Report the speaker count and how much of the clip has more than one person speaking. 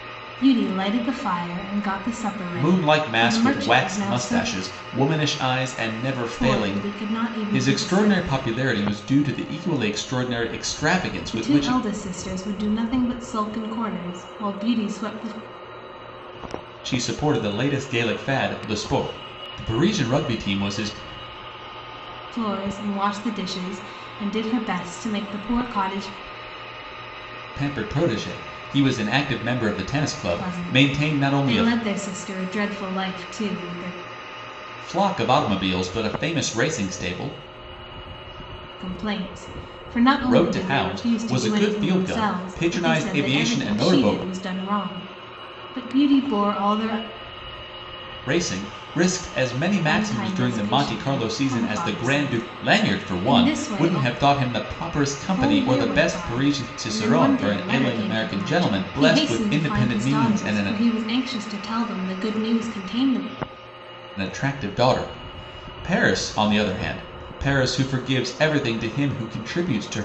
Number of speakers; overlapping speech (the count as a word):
two, about 27%